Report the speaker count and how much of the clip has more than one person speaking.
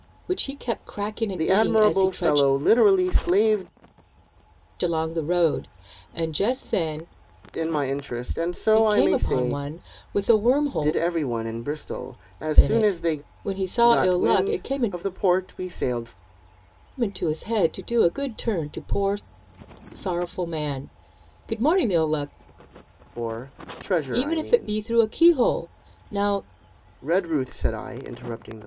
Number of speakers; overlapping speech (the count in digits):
2, about 17%